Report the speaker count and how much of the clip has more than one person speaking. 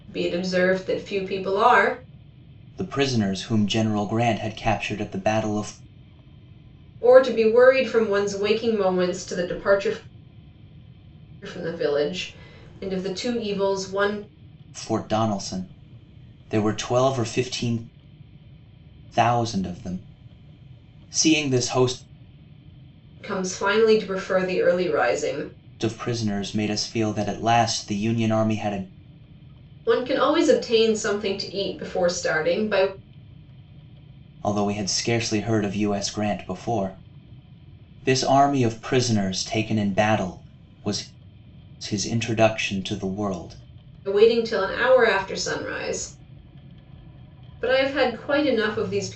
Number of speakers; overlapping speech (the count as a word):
two, no overlap